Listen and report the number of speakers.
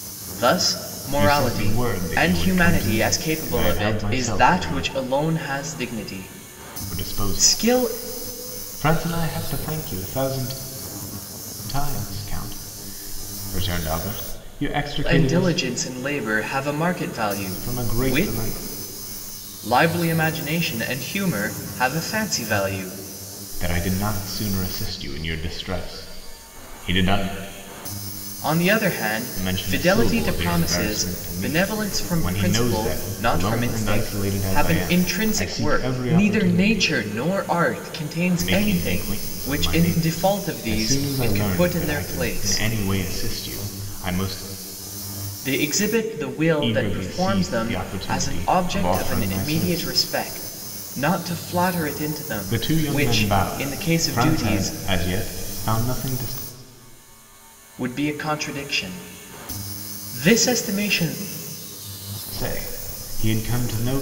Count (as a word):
two